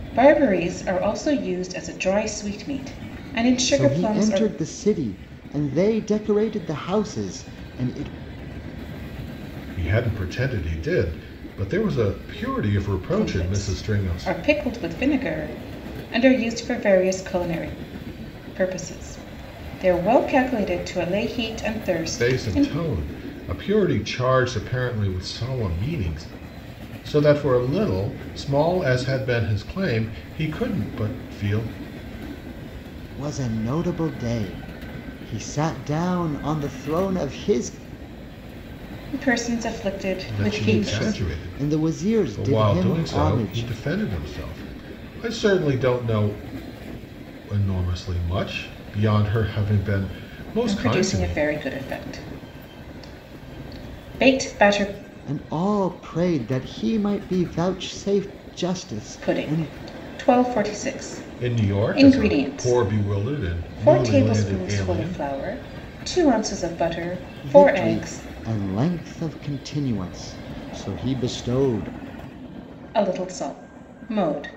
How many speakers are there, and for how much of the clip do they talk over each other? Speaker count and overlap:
3, about 14%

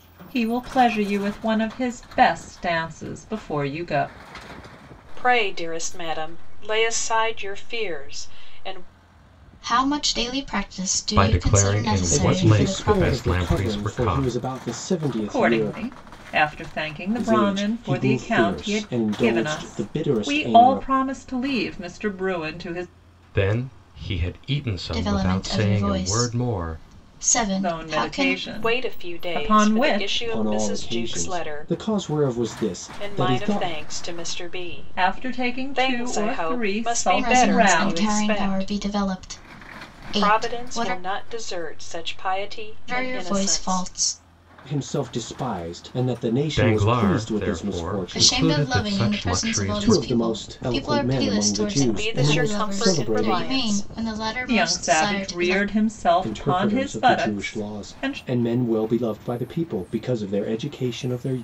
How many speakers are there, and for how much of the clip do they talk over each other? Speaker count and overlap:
5, about 50%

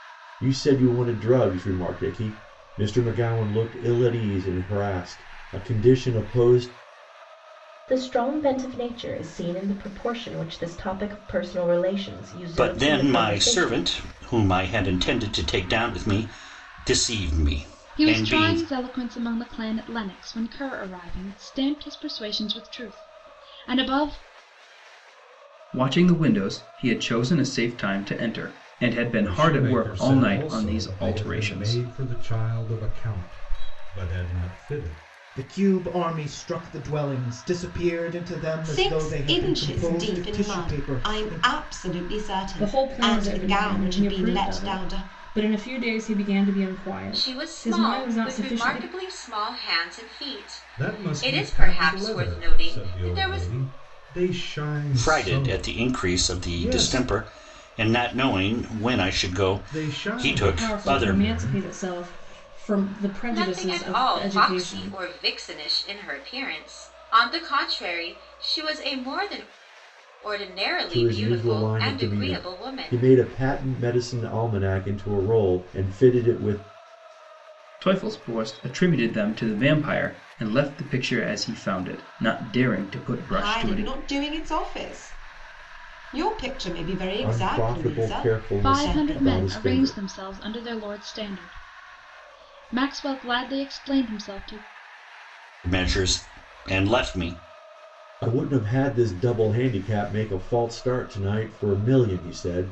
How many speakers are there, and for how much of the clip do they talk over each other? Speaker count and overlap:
10, about 25%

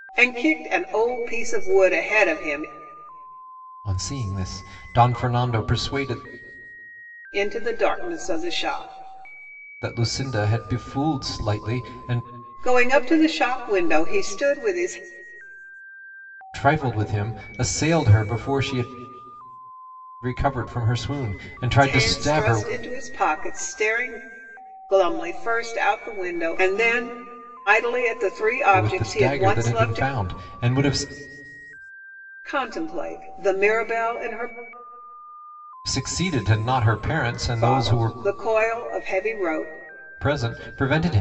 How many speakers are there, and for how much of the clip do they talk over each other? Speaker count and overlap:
2, about 7%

